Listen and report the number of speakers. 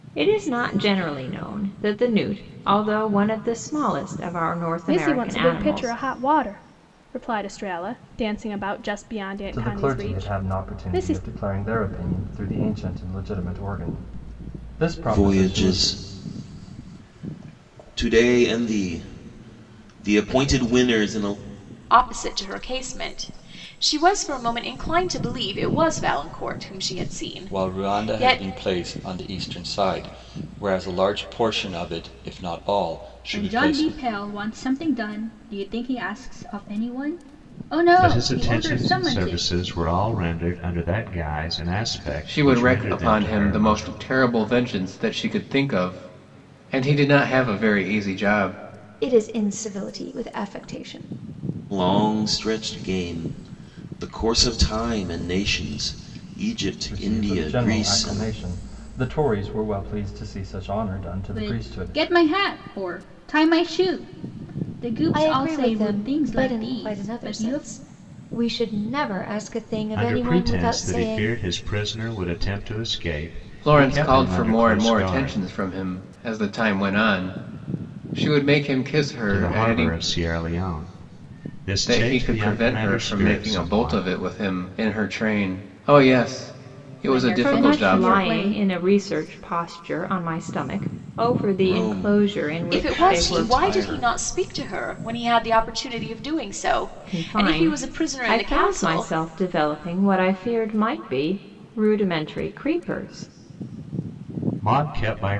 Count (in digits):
10